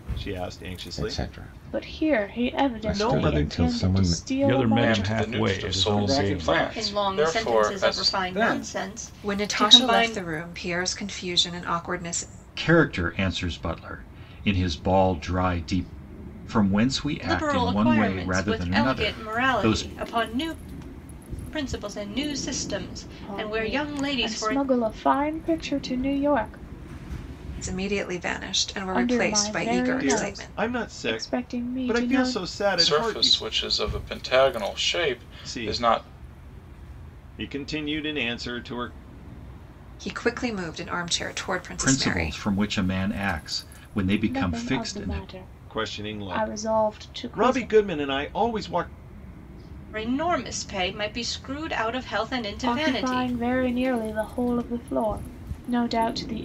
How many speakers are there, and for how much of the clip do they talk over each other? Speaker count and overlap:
9, about 39%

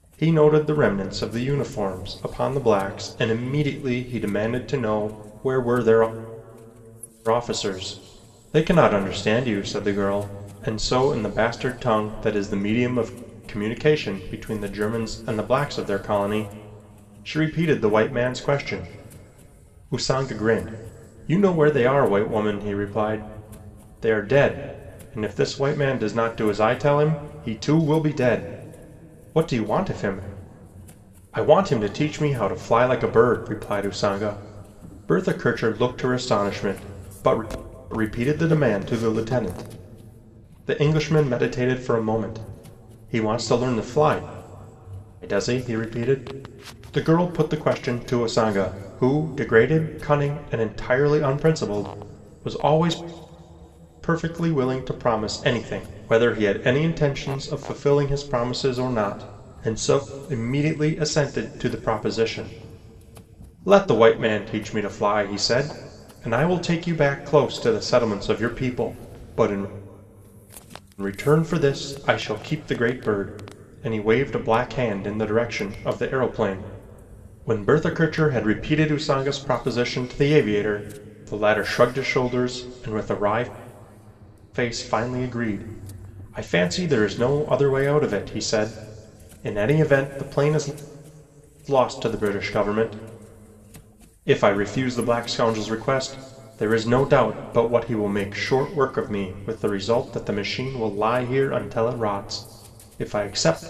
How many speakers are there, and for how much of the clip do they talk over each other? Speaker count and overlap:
1, no overlap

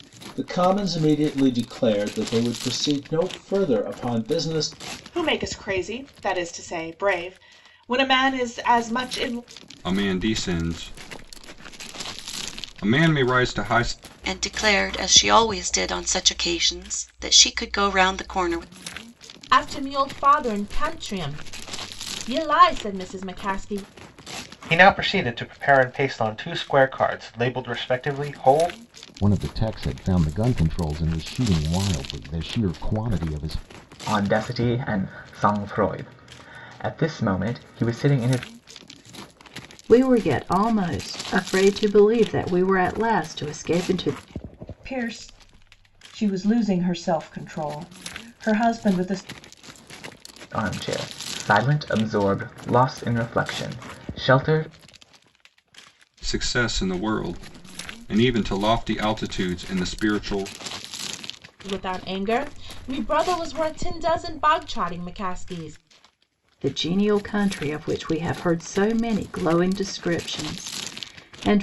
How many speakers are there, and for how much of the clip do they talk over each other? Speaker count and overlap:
10, no overlap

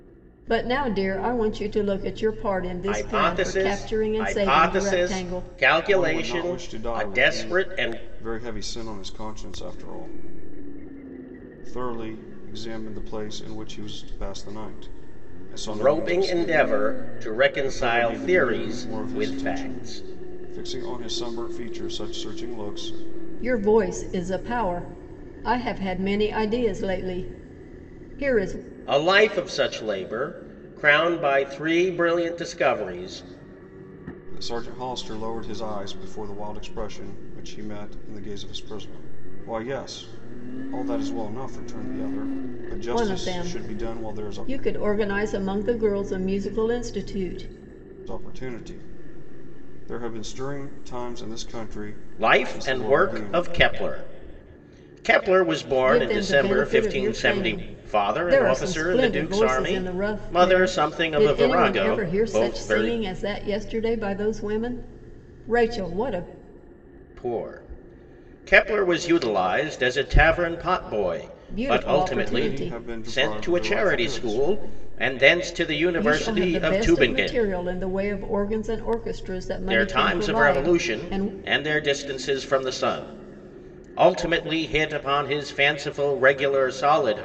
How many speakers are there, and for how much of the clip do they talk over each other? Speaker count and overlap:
3, about 27%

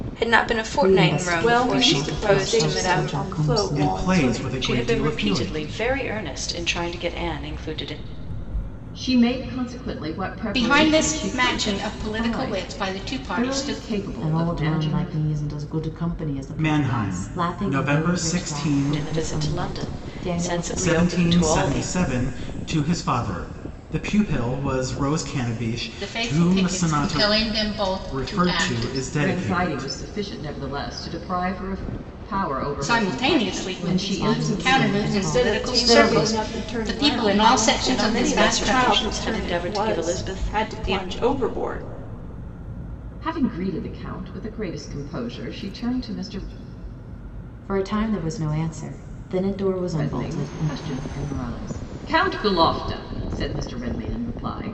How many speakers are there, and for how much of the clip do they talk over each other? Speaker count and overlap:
7, about 49%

